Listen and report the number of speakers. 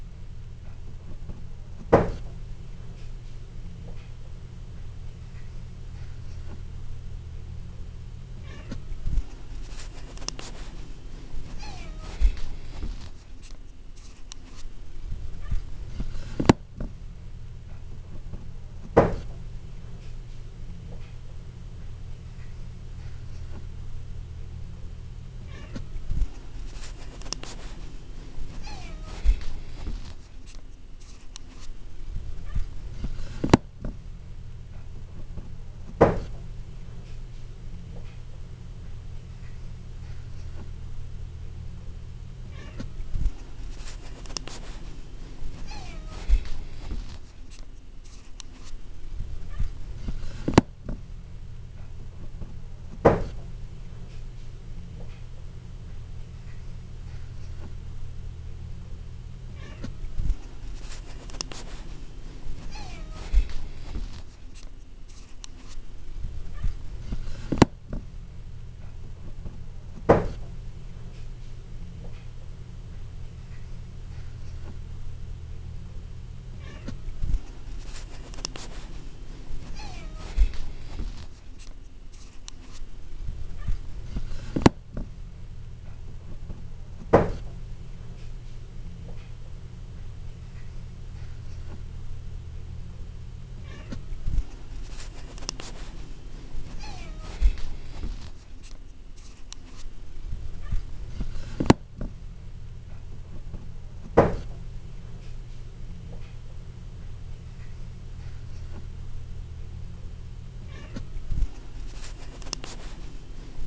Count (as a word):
zero